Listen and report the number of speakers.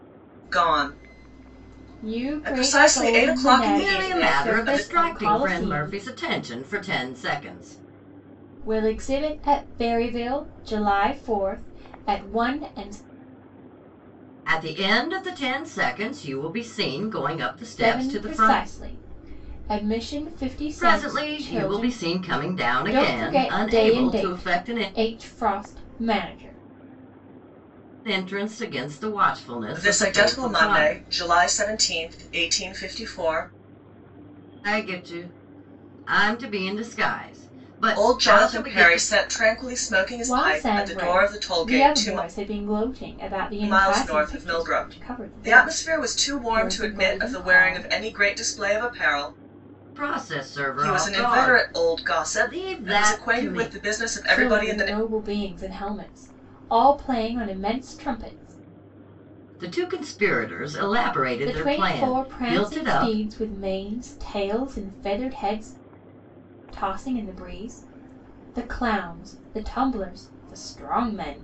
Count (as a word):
three